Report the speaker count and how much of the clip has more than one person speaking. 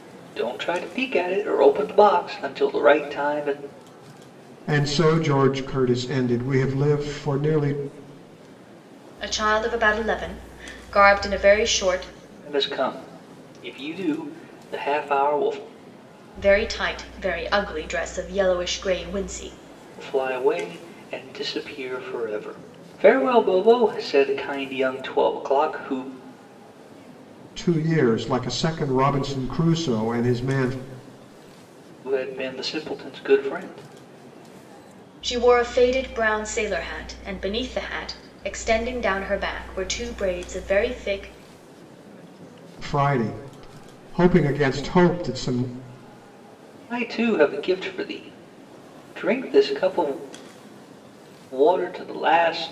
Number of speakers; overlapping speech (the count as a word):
three, no overlap